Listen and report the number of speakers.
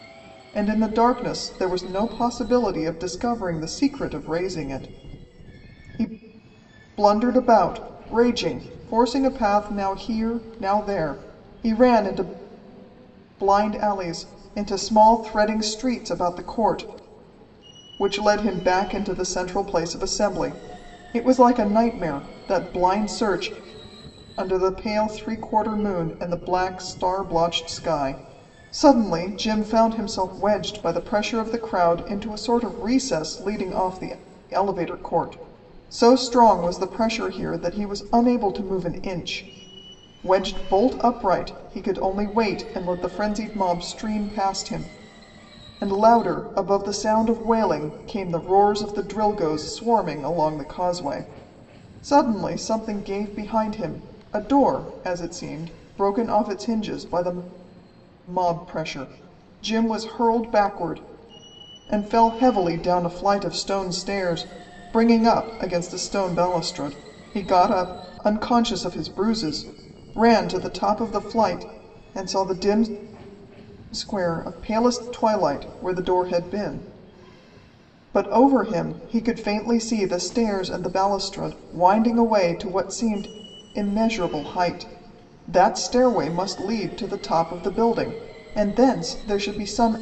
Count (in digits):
1